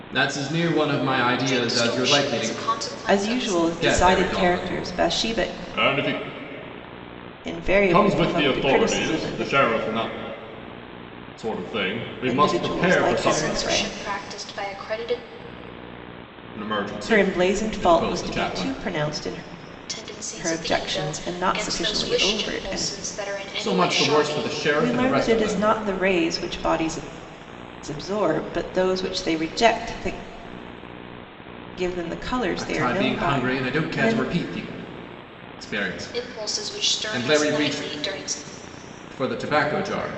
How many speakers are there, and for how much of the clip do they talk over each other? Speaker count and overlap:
three, about 41%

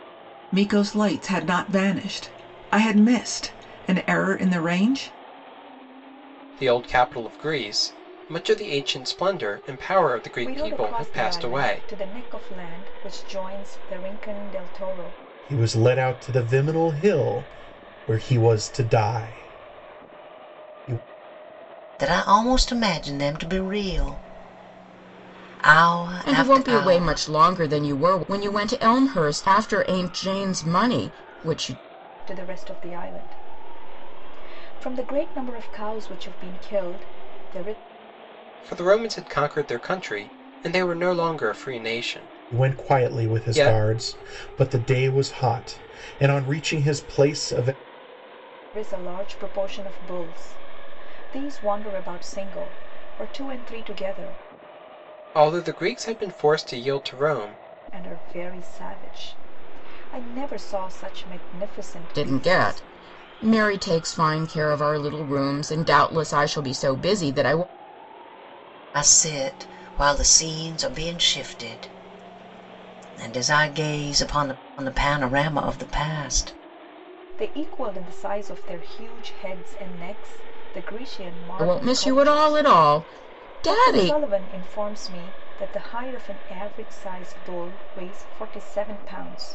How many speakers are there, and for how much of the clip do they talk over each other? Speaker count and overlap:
six, about 7%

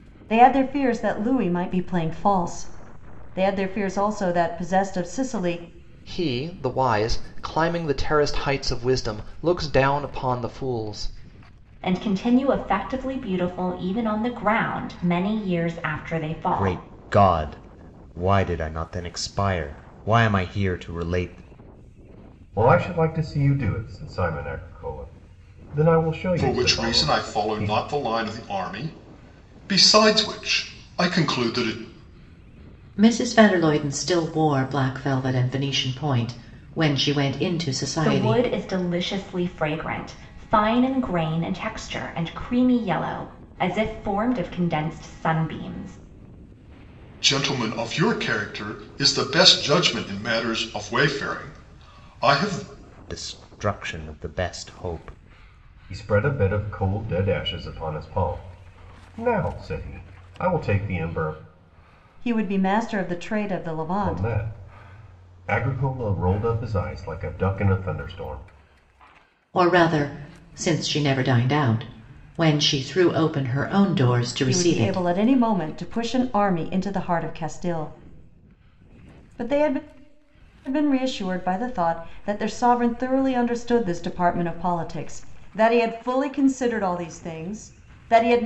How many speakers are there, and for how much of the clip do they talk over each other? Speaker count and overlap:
seven, about 4%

